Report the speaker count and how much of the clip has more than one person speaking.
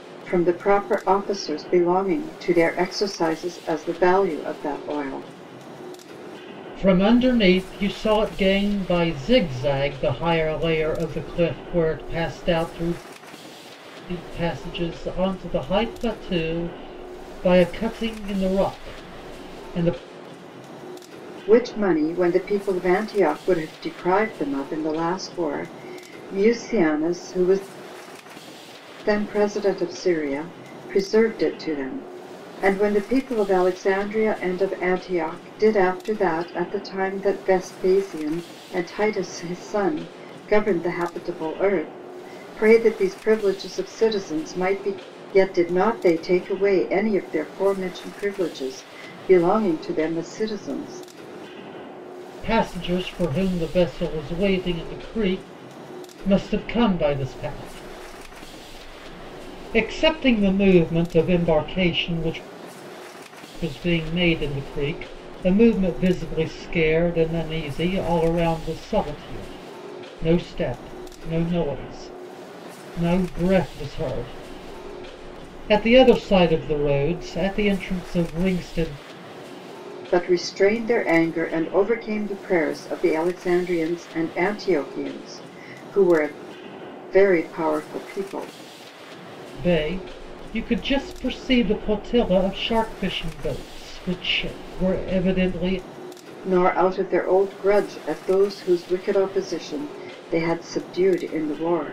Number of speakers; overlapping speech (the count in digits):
2, no overlap